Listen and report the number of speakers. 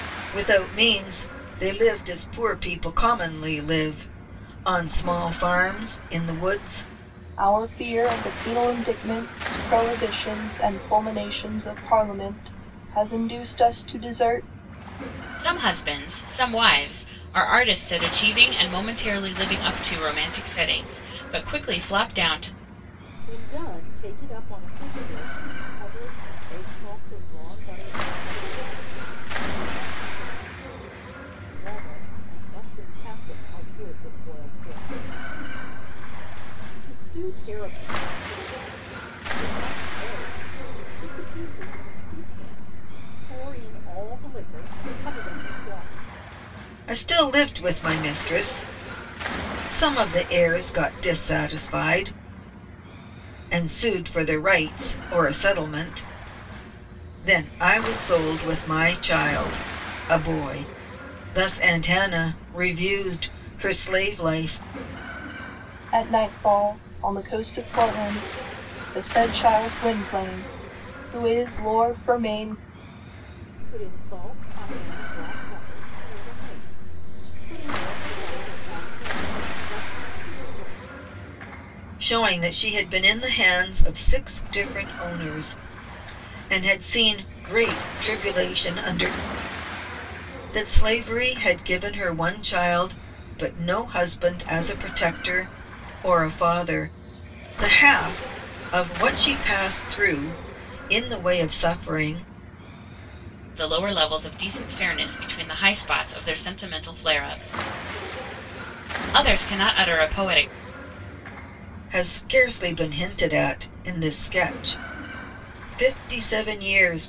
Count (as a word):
four